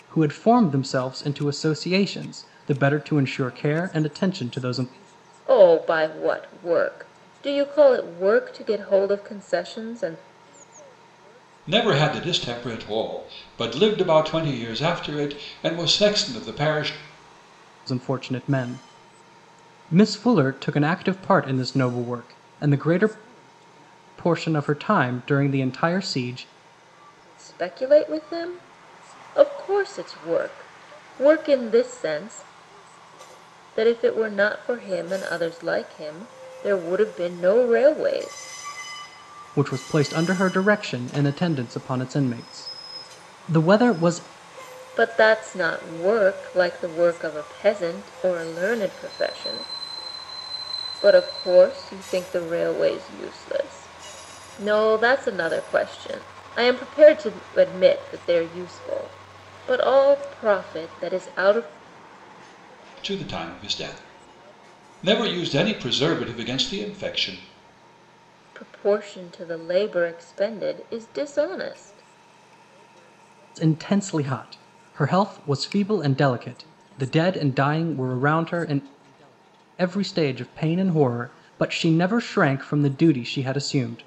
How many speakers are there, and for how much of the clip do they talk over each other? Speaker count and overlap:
three, no overlap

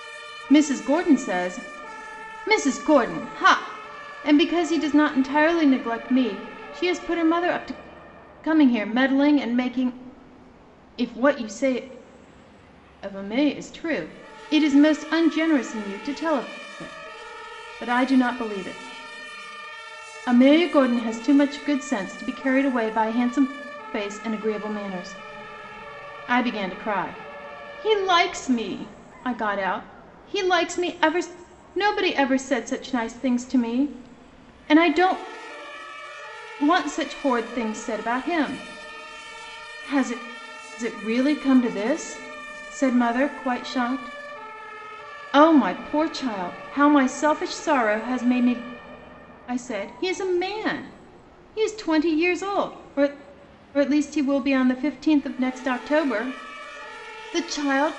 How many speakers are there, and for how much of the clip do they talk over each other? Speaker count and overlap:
one, no overlap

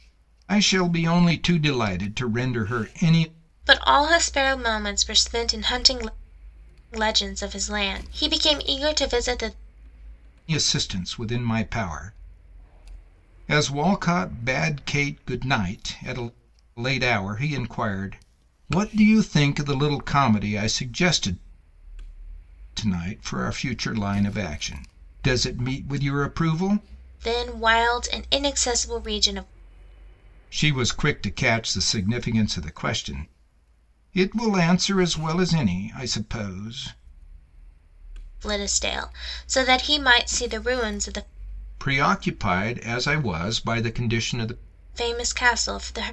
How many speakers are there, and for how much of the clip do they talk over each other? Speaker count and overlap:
two, no overlap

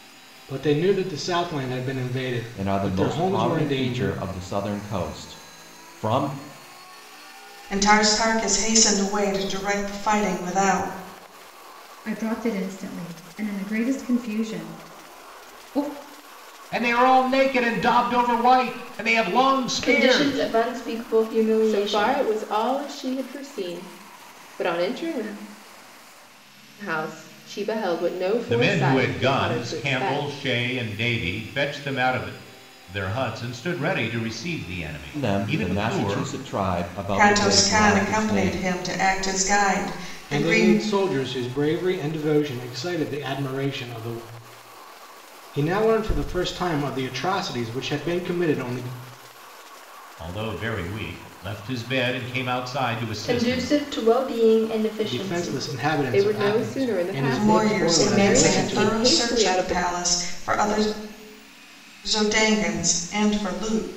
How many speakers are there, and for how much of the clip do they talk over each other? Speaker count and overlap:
seven, about 21%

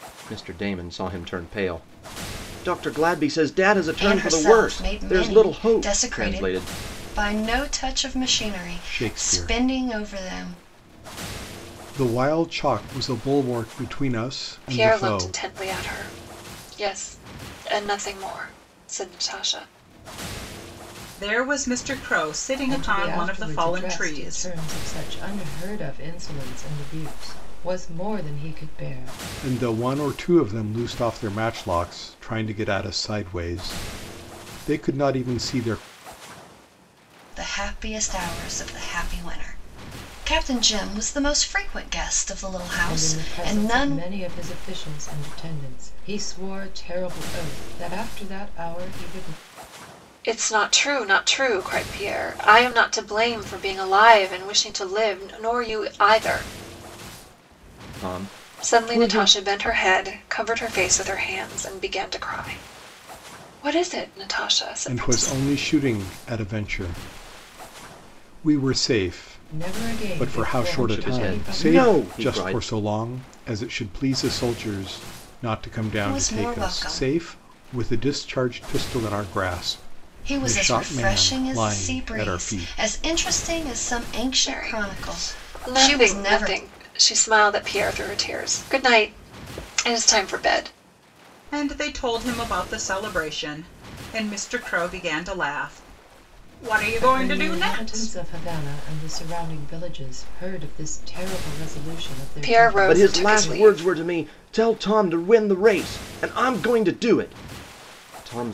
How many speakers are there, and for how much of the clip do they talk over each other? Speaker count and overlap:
six, about 20%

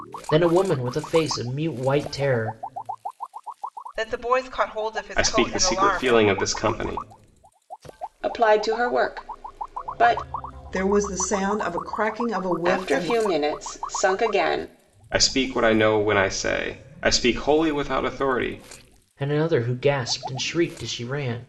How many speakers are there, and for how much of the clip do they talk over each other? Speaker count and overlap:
five, about 8%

